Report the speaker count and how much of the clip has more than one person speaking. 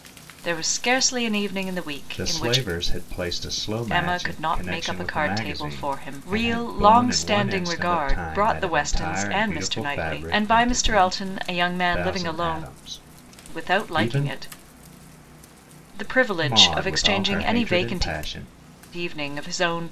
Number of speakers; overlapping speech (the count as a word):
two, about 56%